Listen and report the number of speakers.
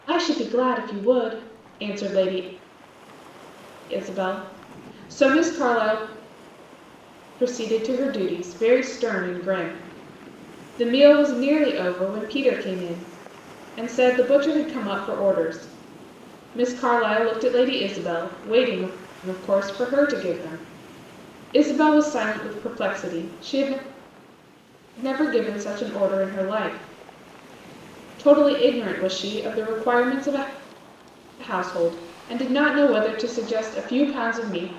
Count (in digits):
1